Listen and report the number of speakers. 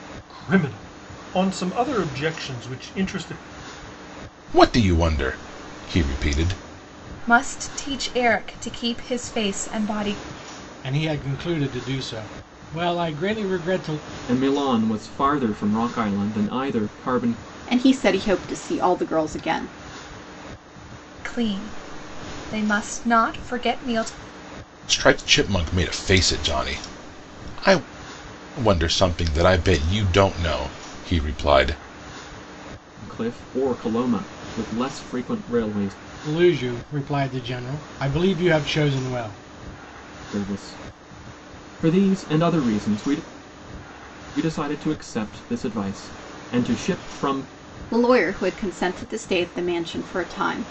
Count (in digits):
6